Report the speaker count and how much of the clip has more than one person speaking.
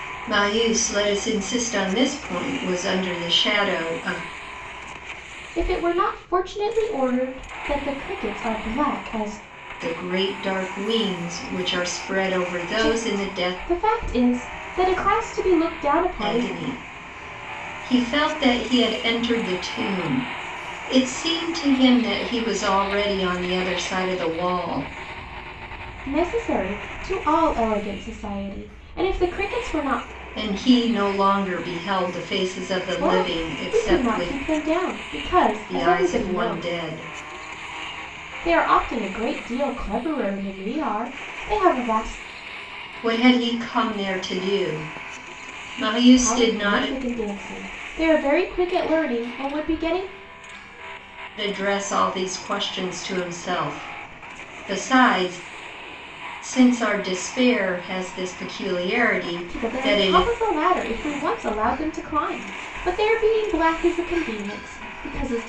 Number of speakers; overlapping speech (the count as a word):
two, about 9%